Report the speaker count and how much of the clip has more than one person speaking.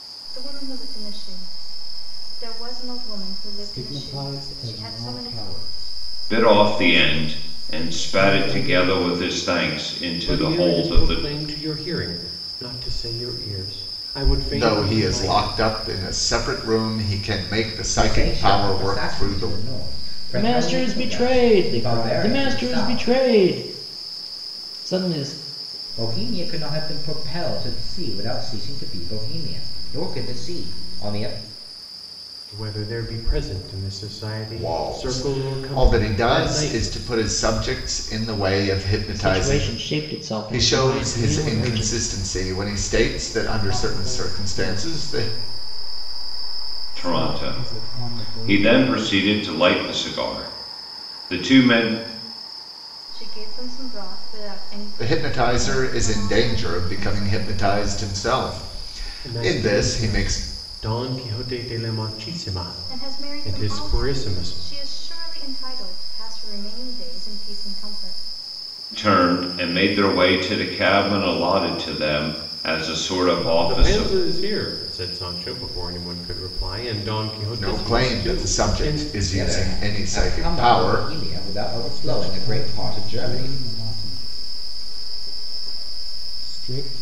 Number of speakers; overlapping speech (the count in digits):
7, about 36%